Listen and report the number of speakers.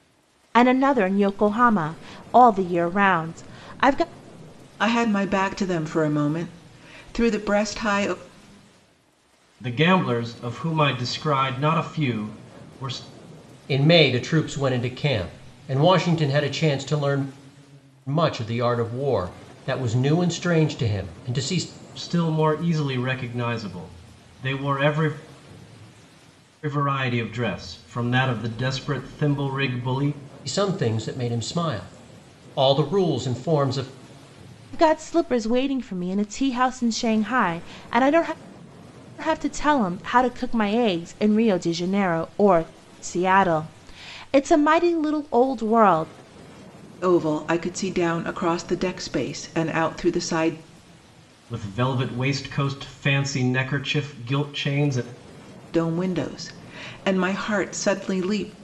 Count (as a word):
four